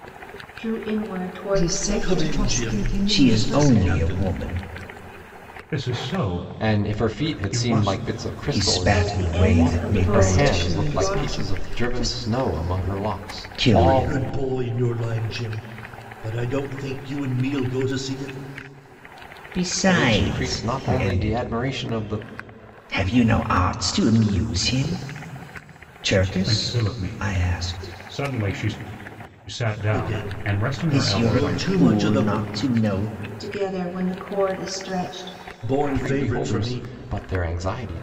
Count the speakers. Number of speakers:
6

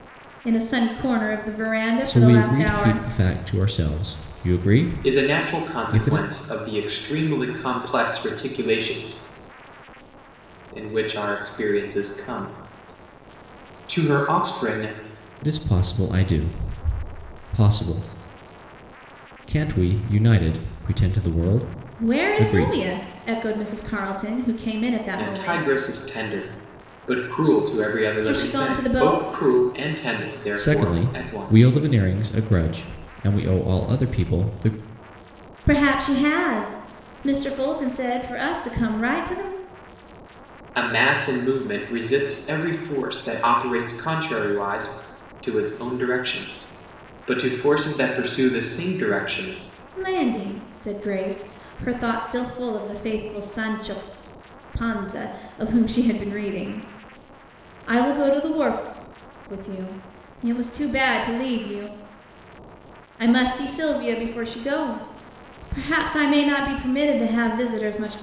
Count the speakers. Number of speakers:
3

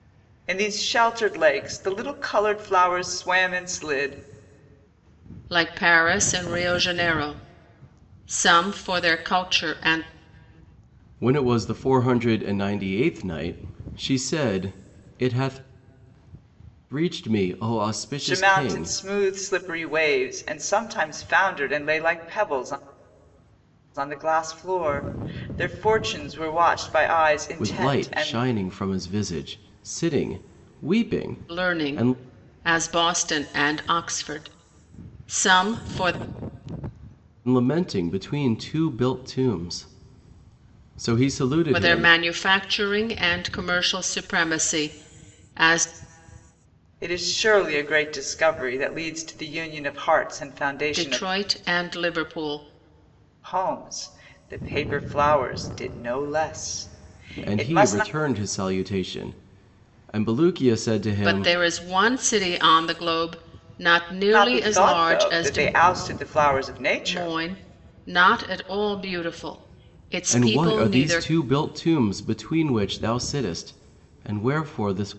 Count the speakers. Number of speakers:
3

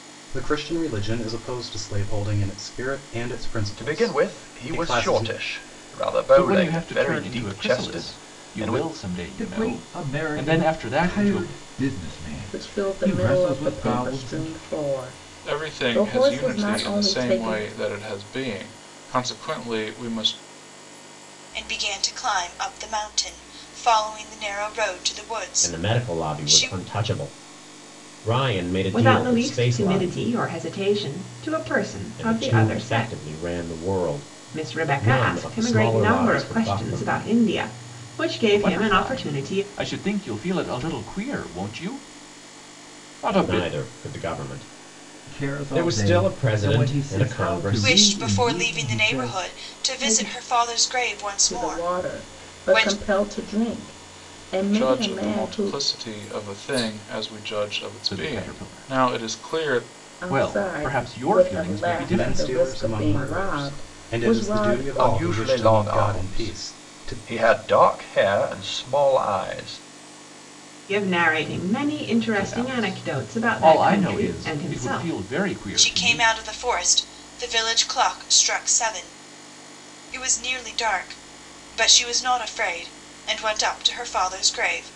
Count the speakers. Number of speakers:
9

